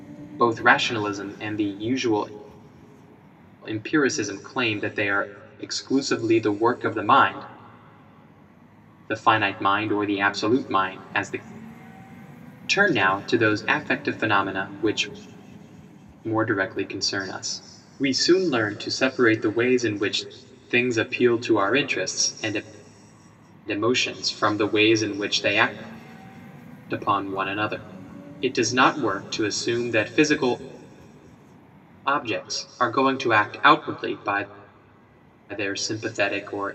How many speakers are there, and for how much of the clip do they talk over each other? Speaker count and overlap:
one, no overlap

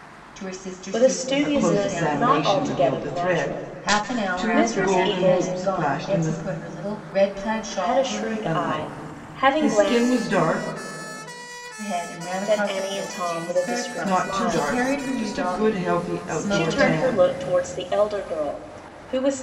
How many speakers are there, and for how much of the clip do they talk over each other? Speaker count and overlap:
three, about 65%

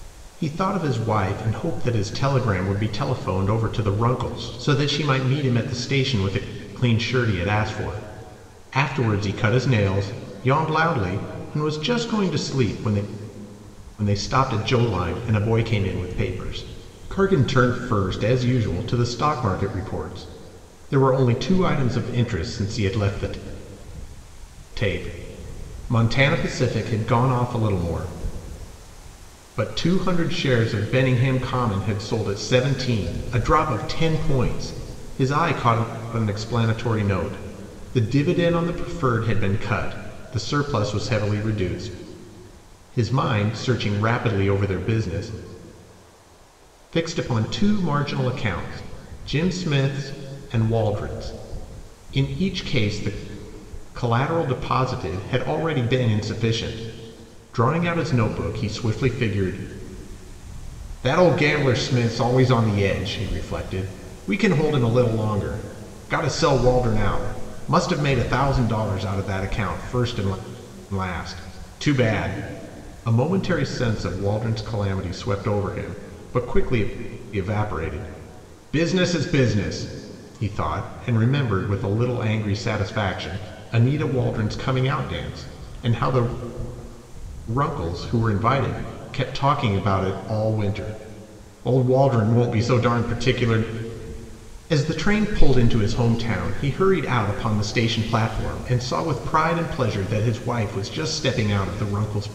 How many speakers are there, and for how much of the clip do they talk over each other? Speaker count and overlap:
one, no overlap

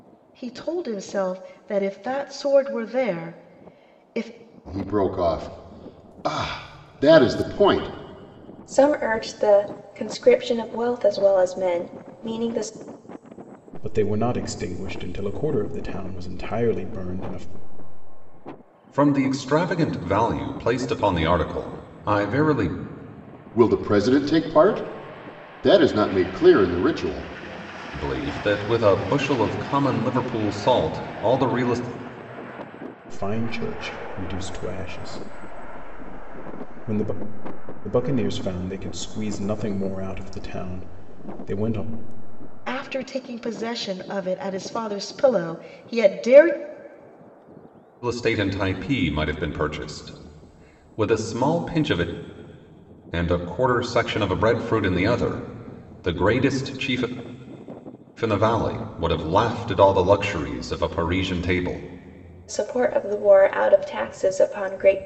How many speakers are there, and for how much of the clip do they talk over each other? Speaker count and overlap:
five, no overlap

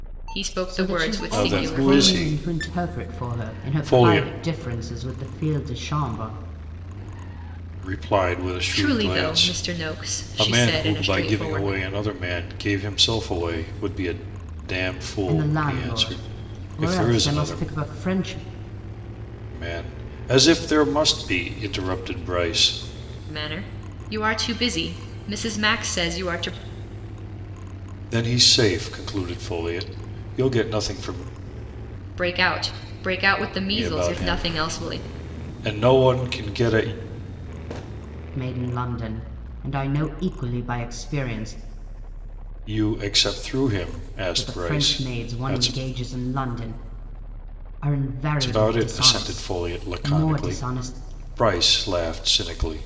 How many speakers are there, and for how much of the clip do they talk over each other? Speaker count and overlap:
three, about 28%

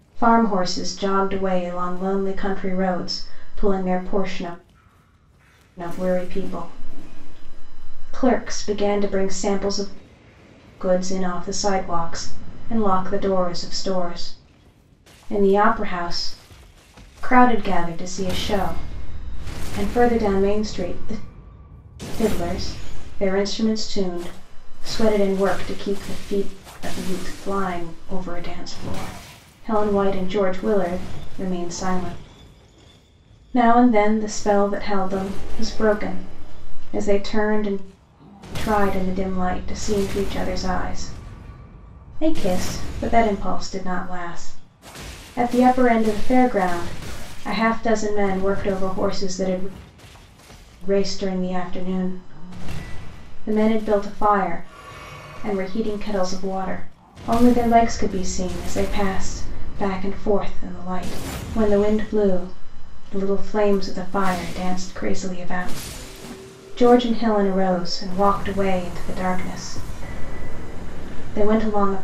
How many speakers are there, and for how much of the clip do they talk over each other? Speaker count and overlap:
one, no overlap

